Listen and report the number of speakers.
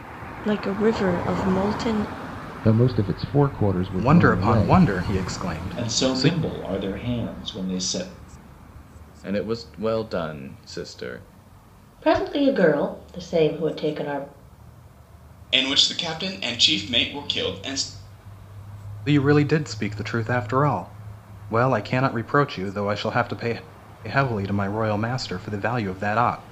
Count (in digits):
7